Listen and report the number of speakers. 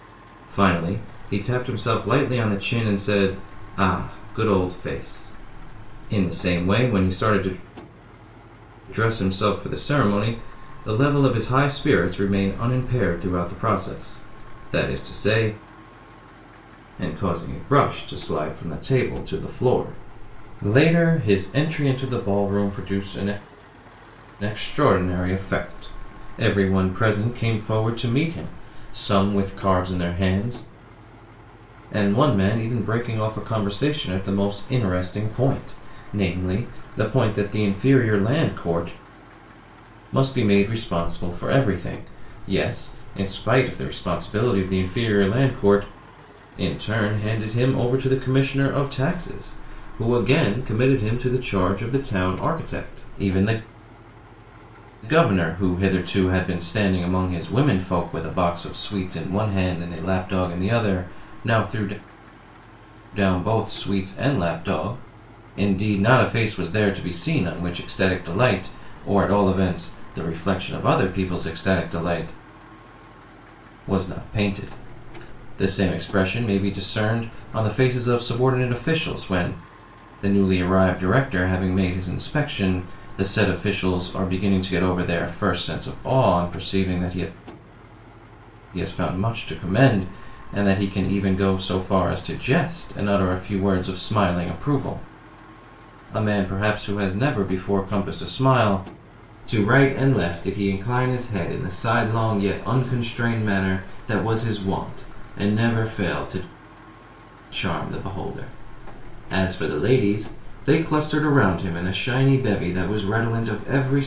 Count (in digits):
1